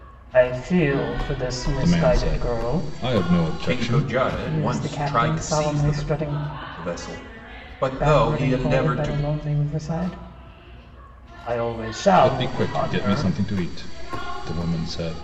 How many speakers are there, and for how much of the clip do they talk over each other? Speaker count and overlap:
three, about 37%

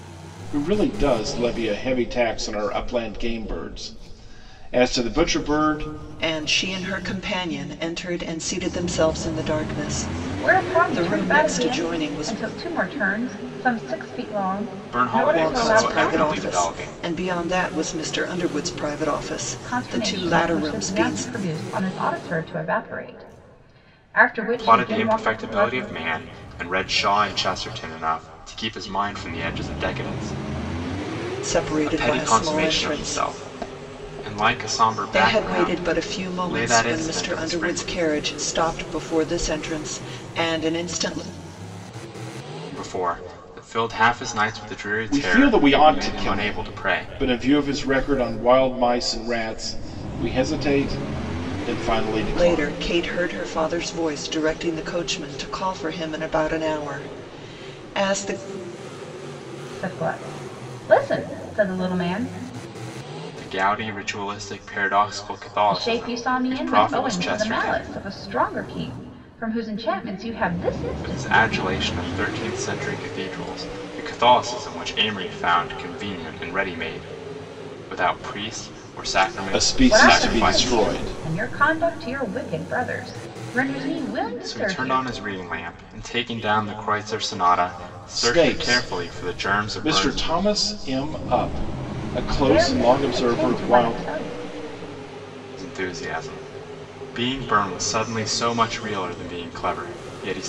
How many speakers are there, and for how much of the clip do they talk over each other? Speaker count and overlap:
four, about 23%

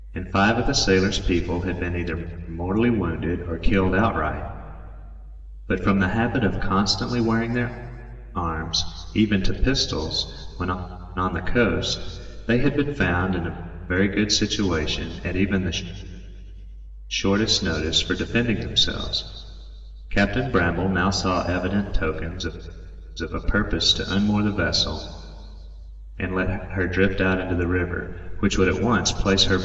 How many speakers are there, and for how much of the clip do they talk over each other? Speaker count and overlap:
one, no overlap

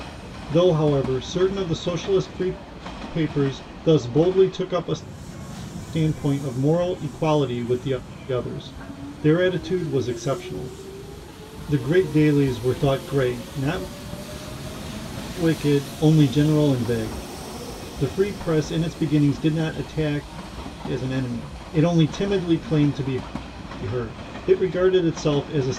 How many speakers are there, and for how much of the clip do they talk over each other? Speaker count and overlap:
one, no overlap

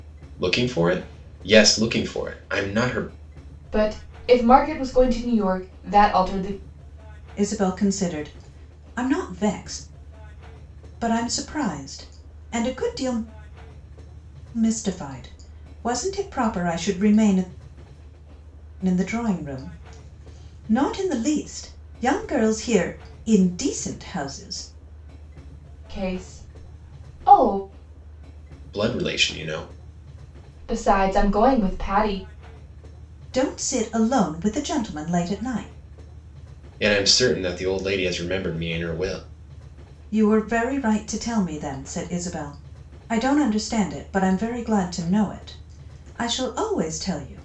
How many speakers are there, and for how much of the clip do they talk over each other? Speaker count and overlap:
three, no overlap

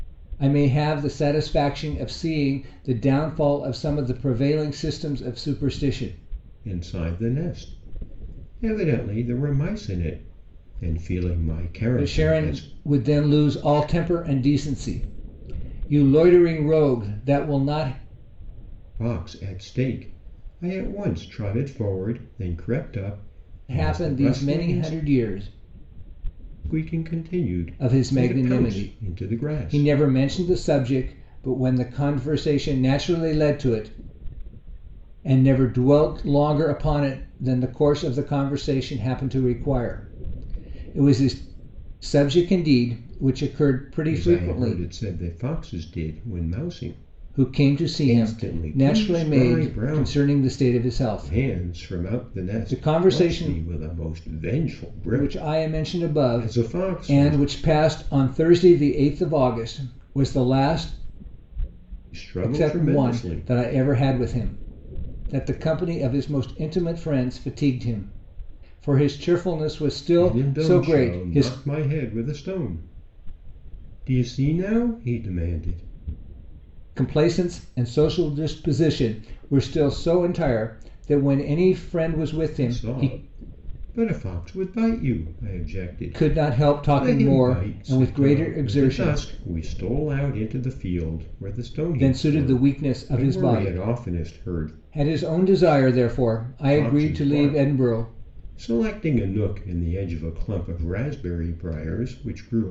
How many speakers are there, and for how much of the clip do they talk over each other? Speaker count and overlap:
two, about 22%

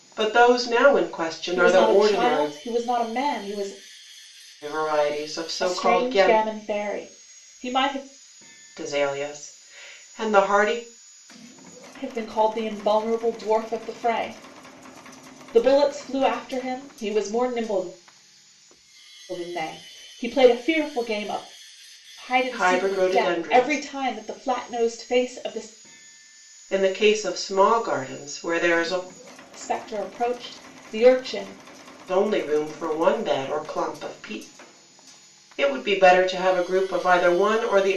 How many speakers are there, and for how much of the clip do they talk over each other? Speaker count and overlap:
two, about 9%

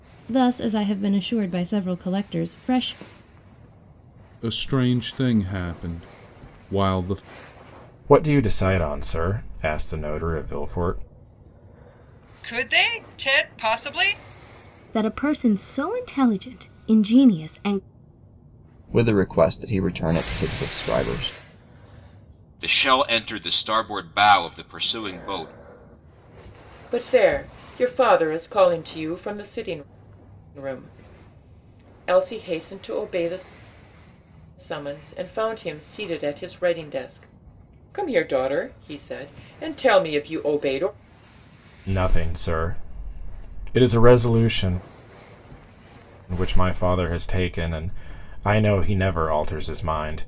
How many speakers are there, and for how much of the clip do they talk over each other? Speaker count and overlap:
eight, no overlap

